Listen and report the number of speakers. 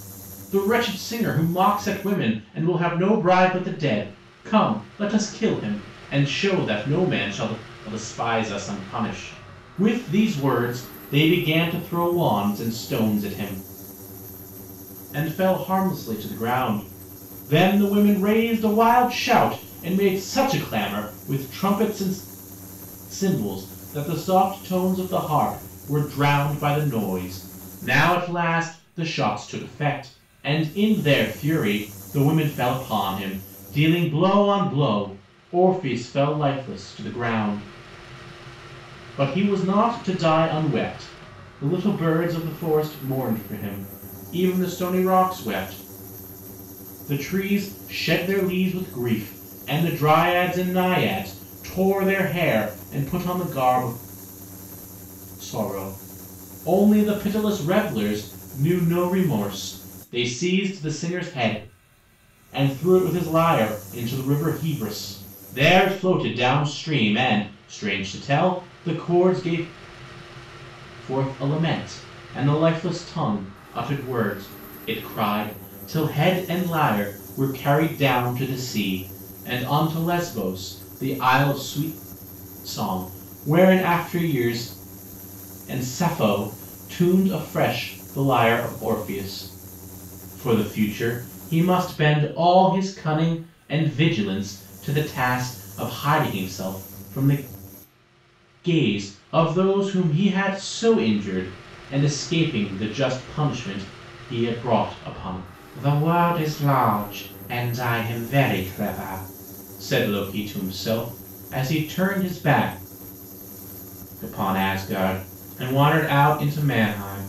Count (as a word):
one